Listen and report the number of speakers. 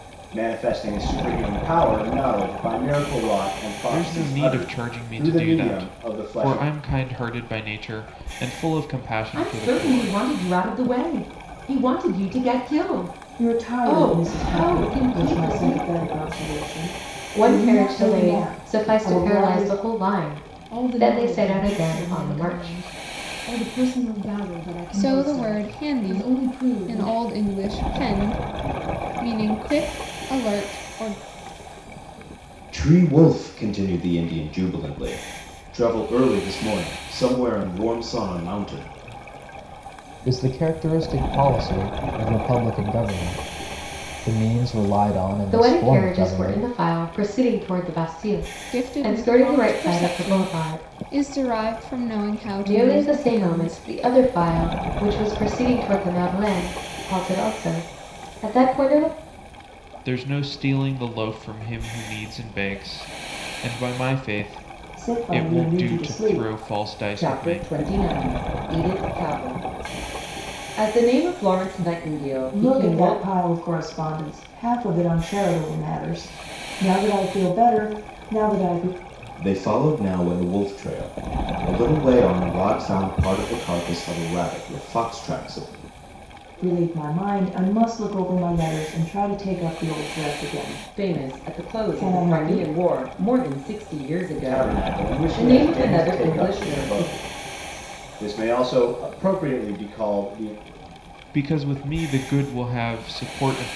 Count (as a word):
nine